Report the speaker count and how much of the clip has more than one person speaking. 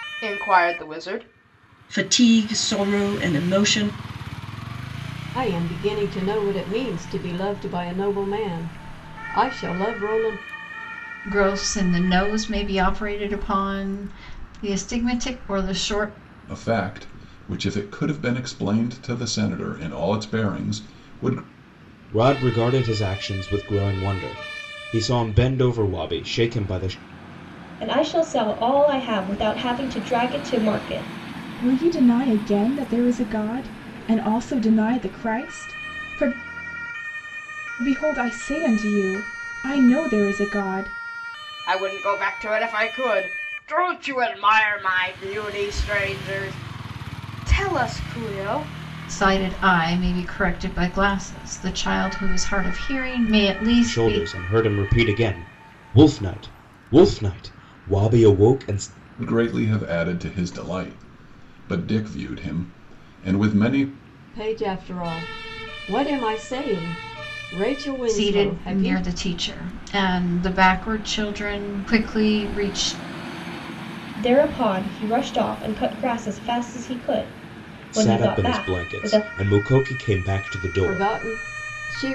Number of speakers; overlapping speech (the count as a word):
eight, about 4%